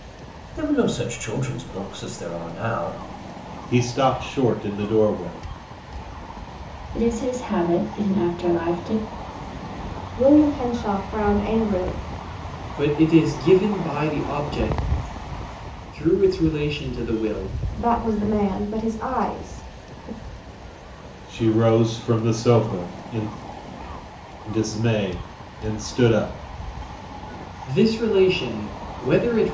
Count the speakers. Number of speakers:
five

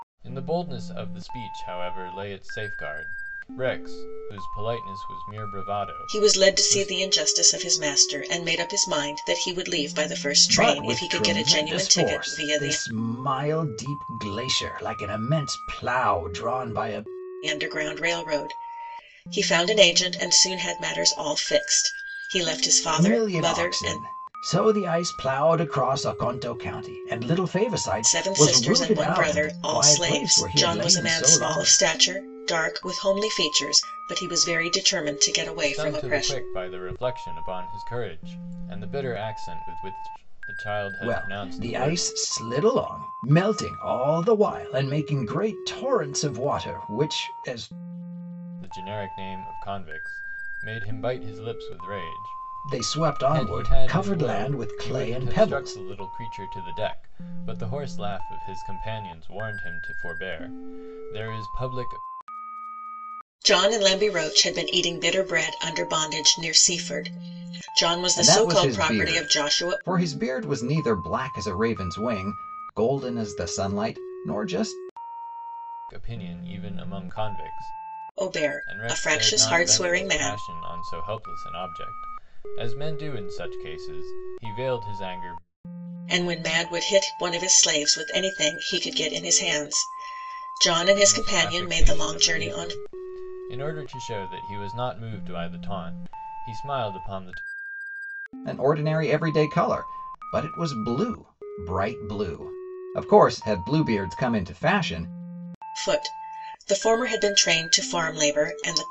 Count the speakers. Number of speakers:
three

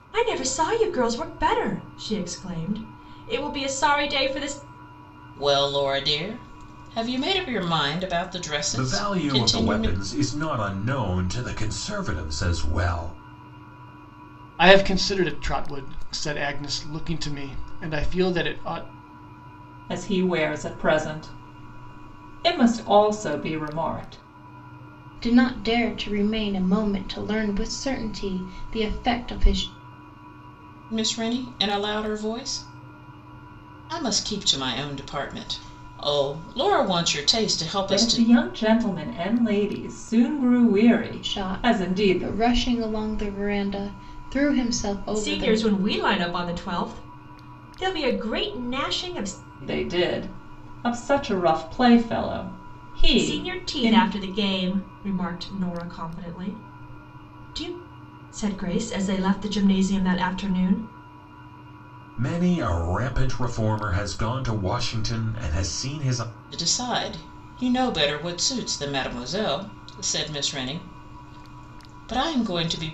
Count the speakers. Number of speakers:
six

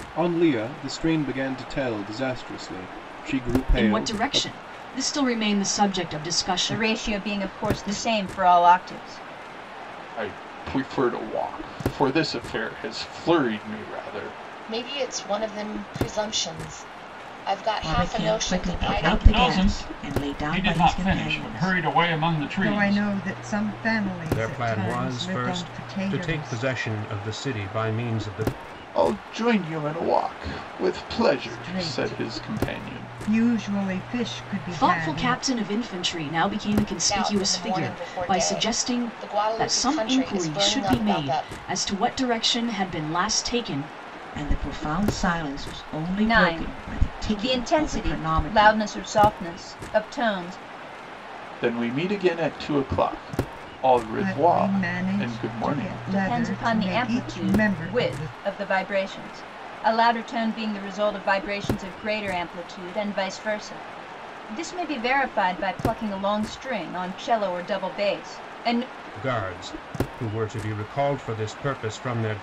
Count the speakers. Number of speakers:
nine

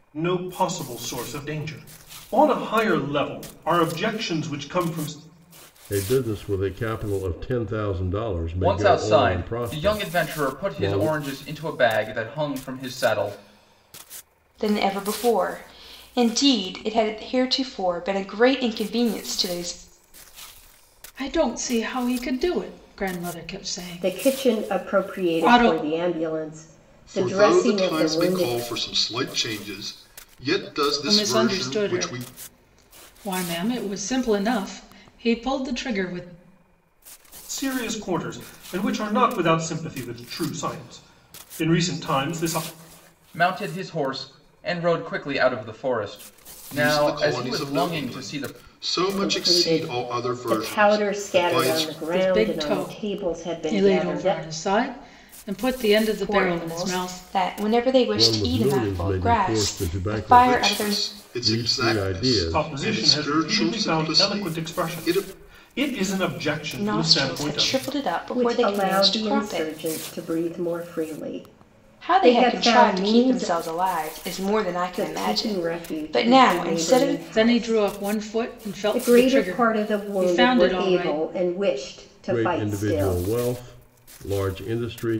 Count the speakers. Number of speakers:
seven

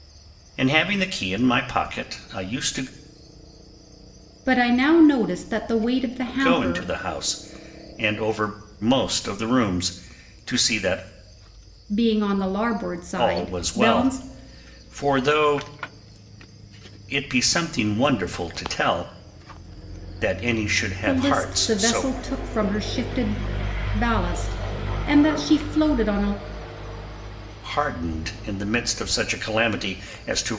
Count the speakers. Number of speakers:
two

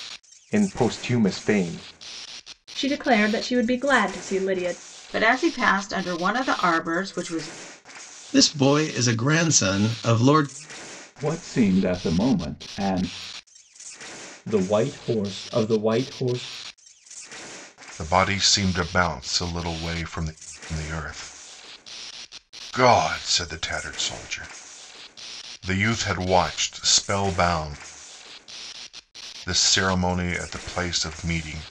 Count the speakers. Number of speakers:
seven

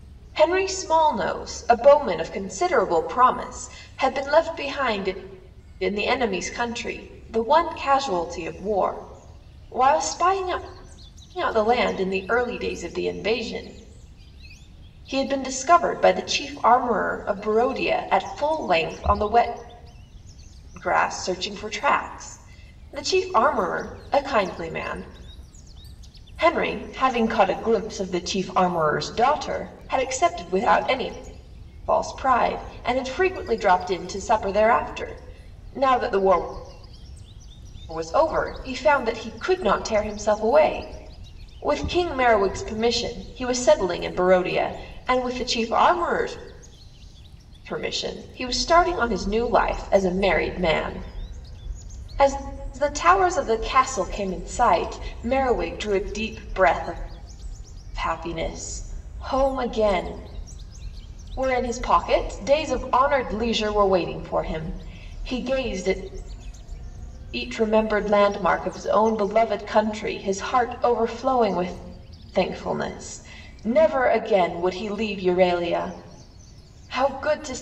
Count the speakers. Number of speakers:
one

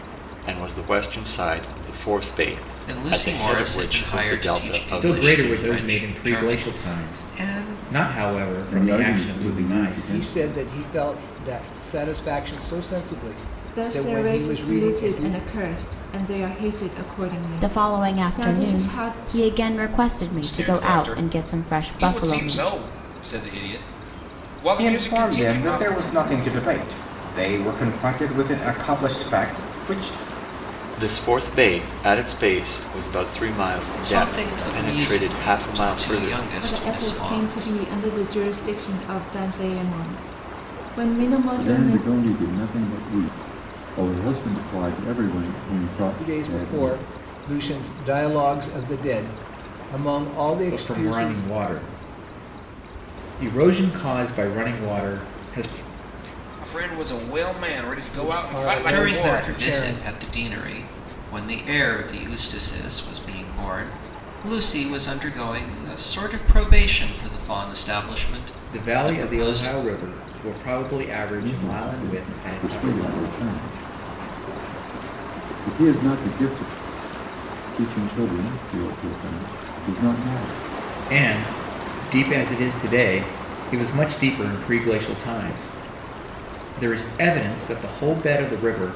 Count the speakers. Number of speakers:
nine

